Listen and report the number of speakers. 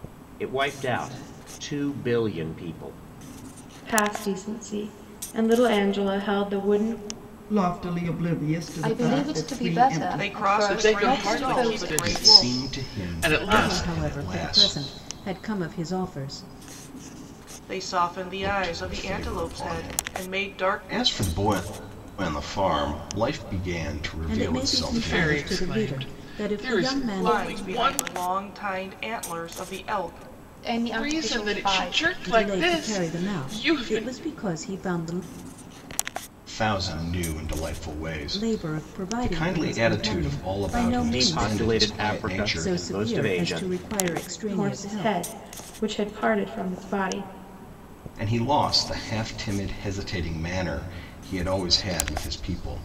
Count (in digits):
8